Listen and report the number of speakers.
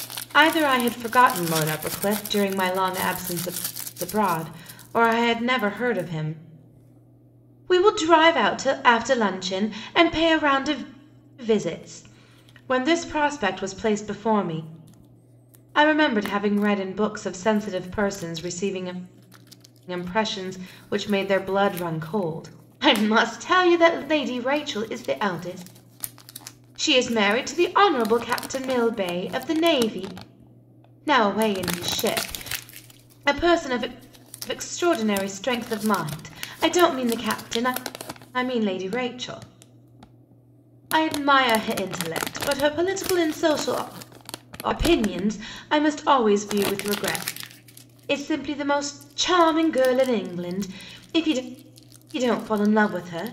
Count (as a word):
one